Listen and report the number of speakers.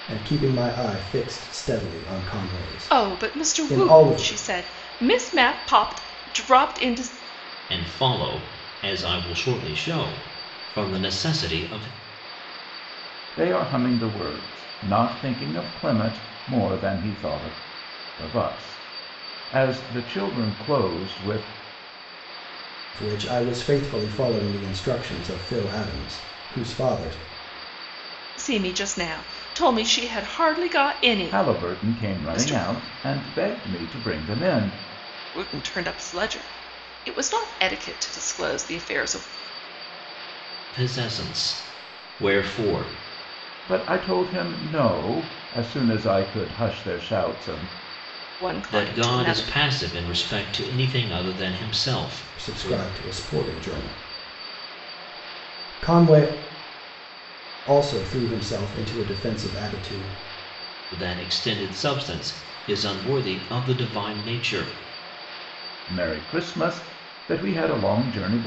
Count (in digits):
4